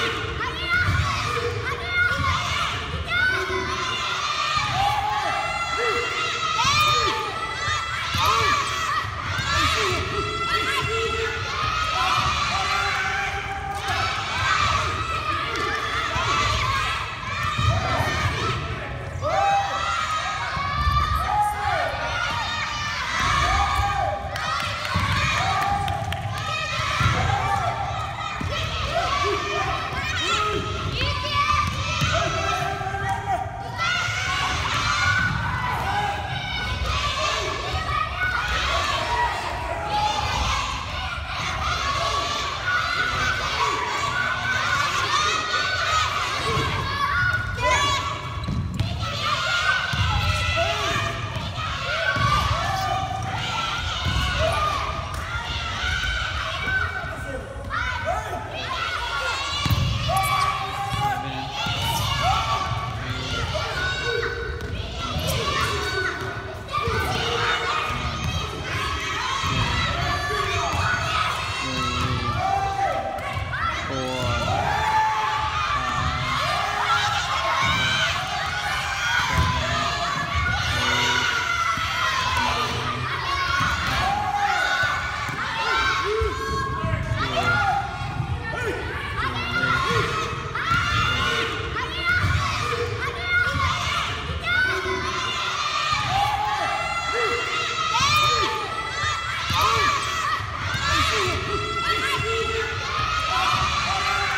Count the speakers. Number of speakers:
0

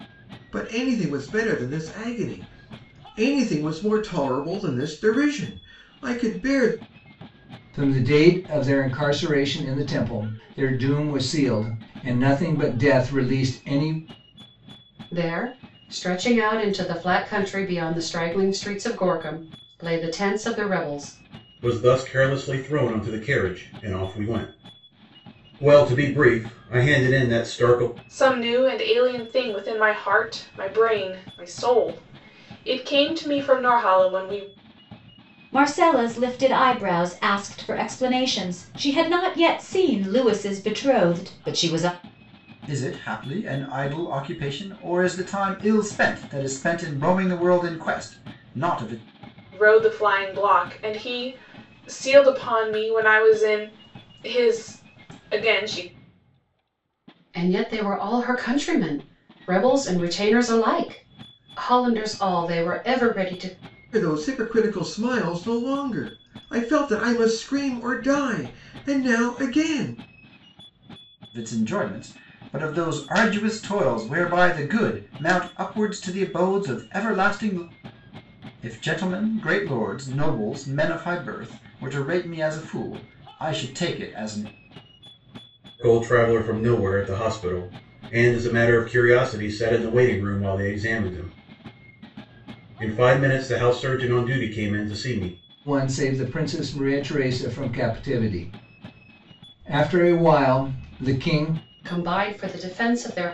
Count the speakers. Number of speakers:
7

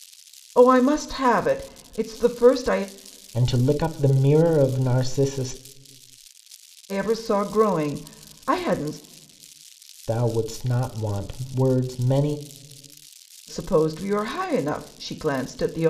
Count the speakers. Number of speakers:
2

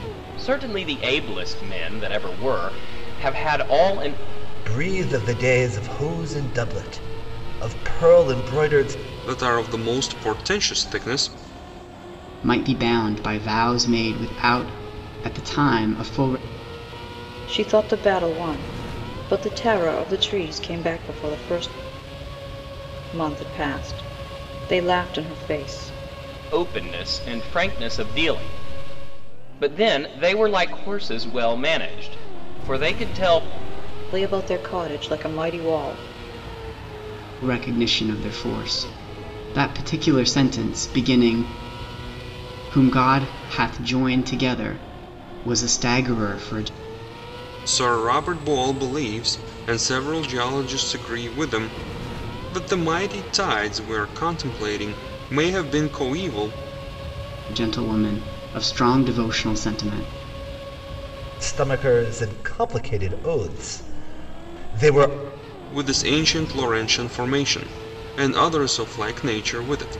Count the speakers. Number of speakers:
5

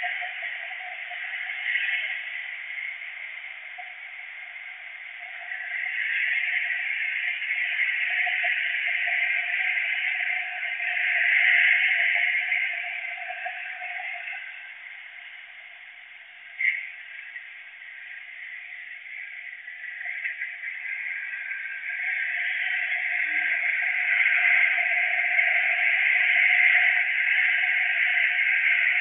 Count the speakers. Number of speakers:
0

